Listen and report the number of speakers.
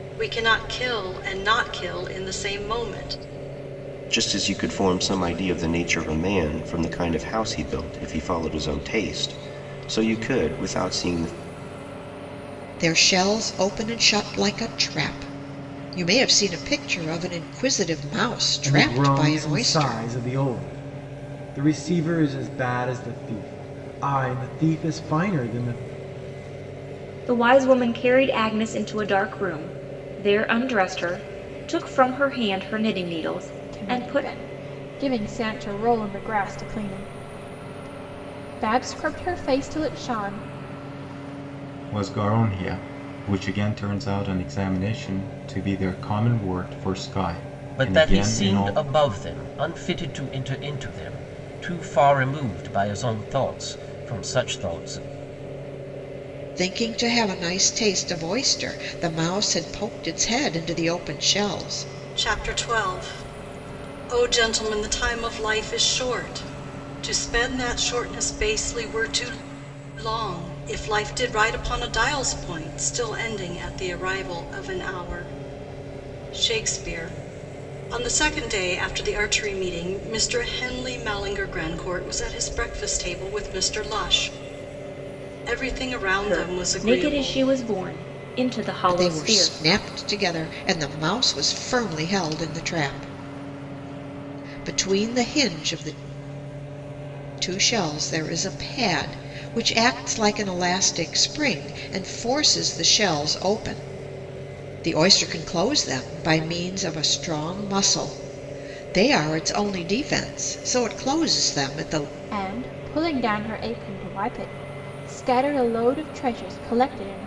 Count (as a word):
eight